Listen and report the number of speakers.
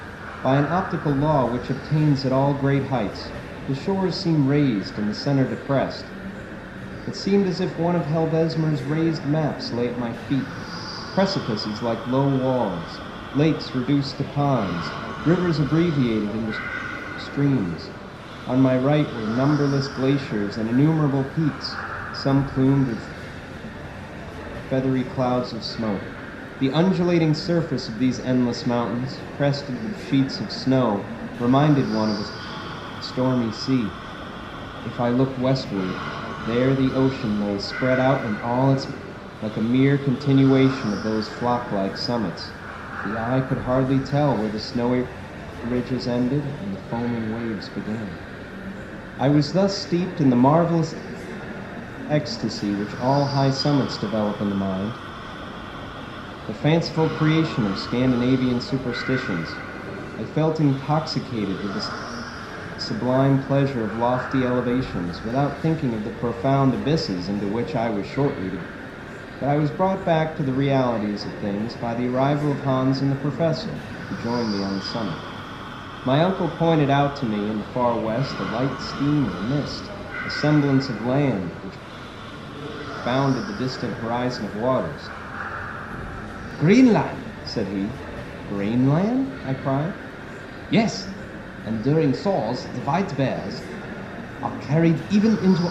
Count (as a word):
one